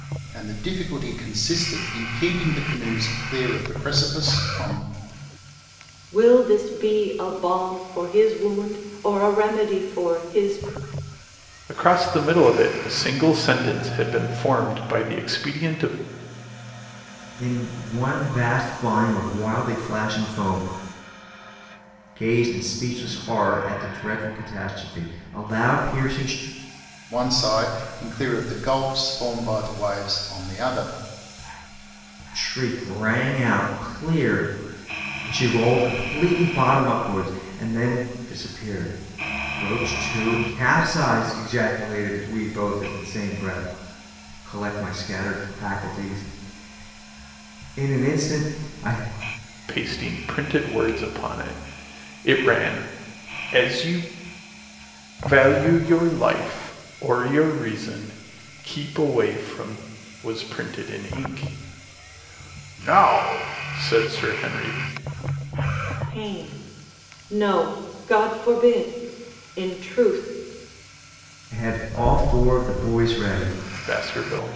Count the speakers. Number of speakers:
4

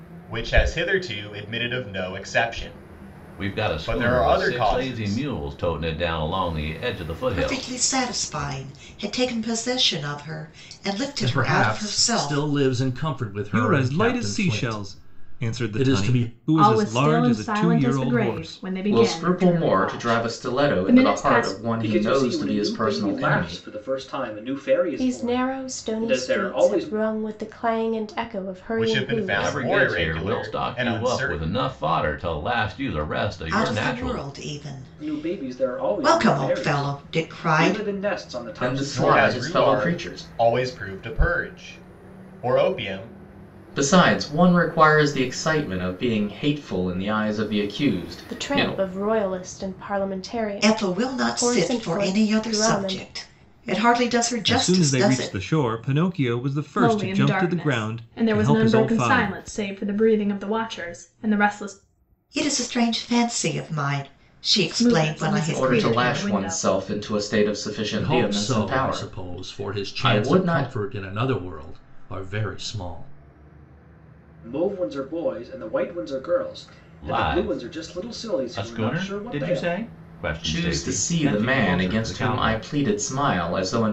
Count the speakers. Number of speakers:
9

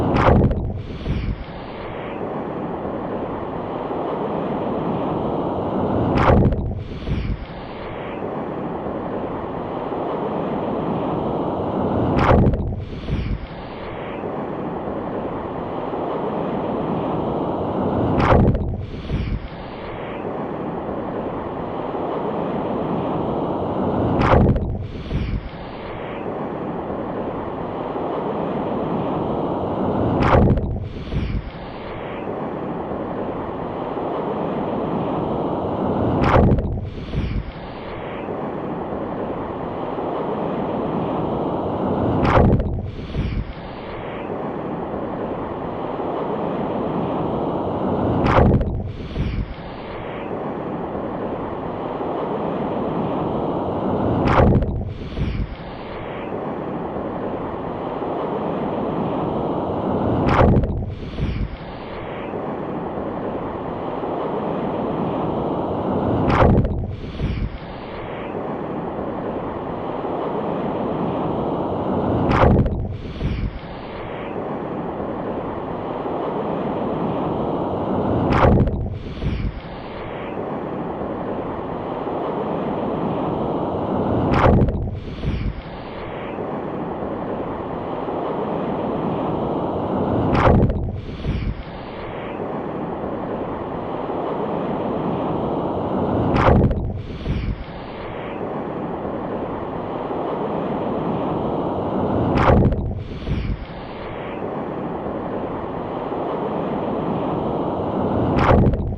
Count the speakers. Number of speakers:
0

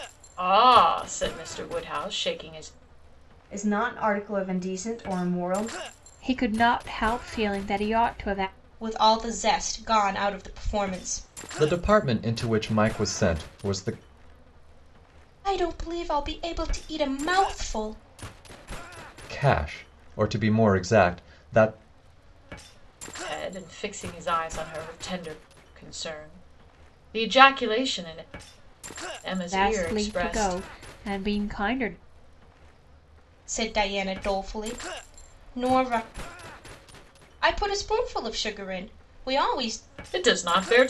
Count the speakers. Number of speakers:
5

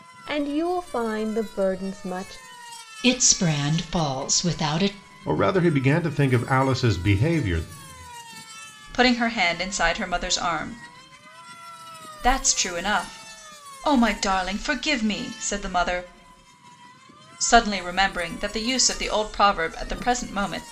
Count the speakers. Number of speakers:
4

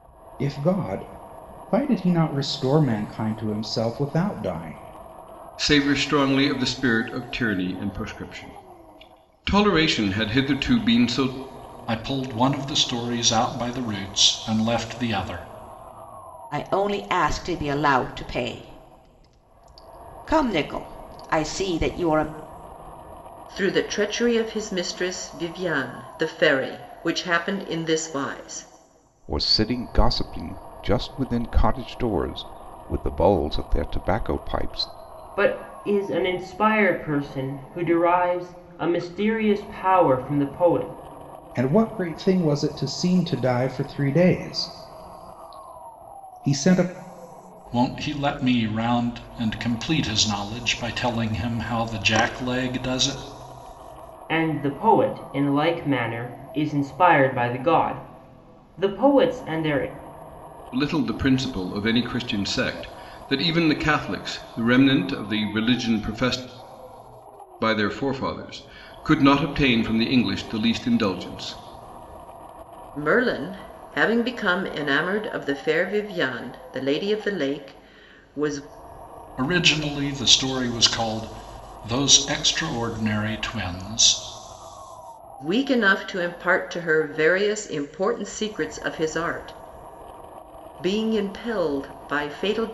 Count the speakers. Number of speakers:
7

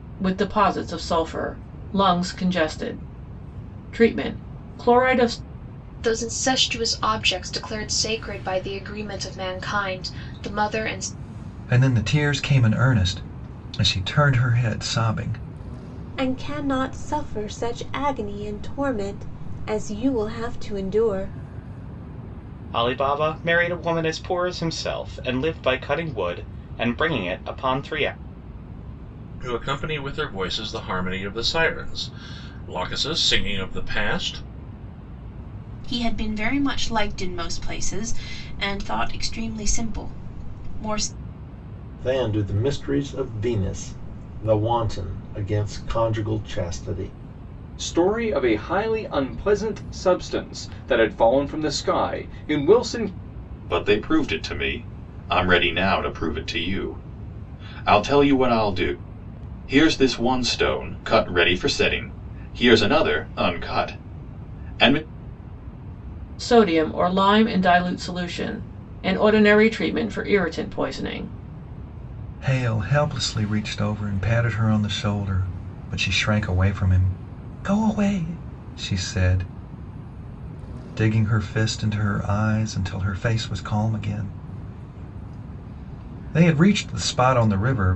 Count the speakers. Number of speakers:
10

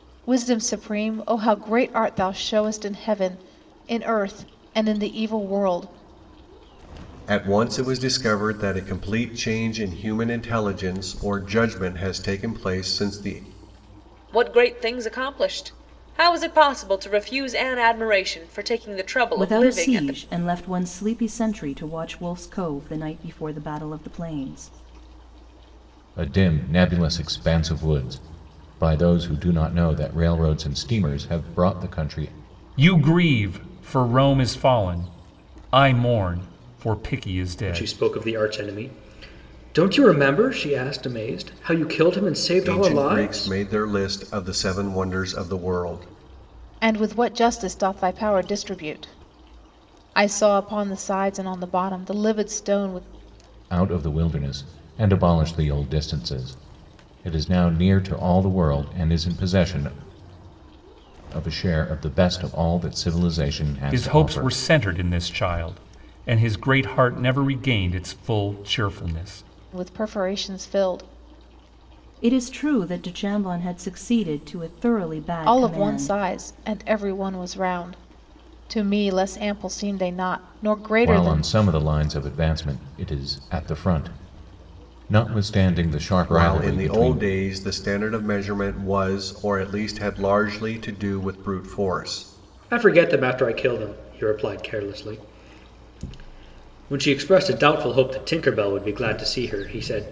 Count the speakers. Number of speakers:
7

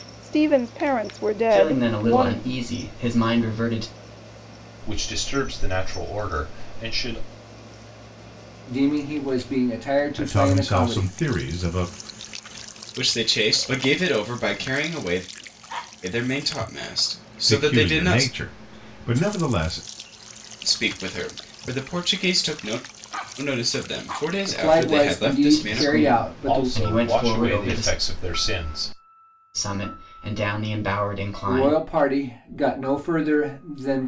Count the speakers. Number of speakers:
6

